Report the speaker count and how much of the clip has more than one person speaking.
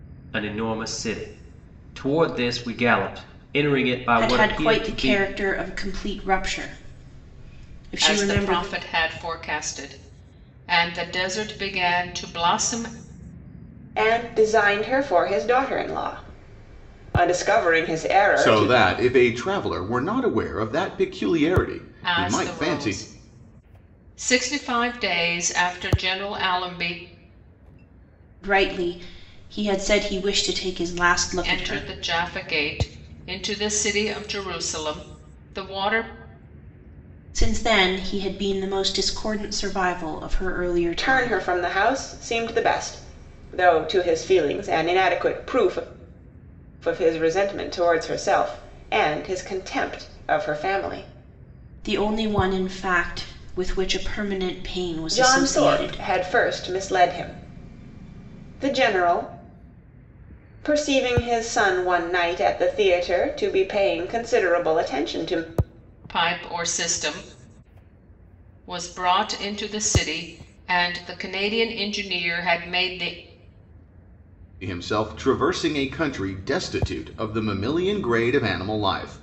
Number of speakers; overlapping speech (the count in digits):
5, about 6%